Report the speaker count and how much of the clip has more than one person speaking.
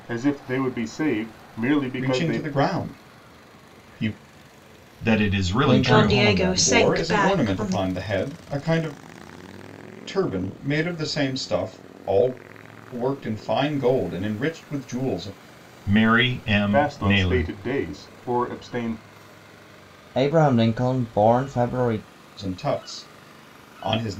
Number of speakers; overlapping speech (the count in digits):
5, about 15%